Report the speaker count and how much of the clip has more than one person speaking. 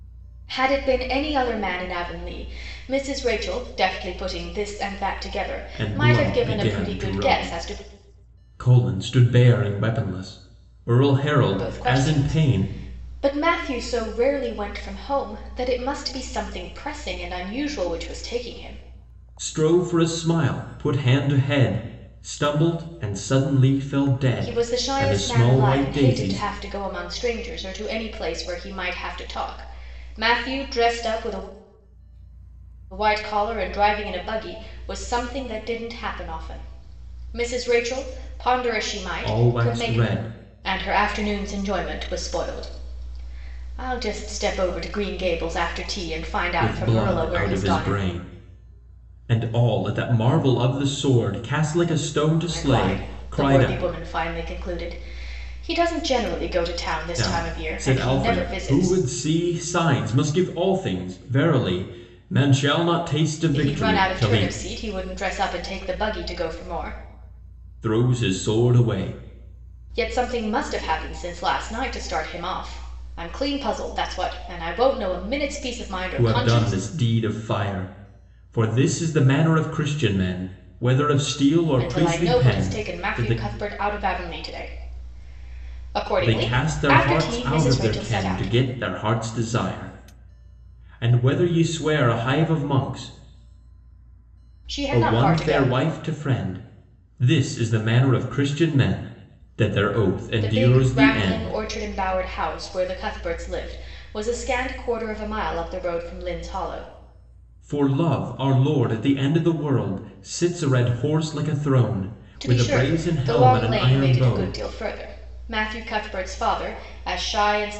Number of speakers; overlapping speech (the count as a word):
two, about 18%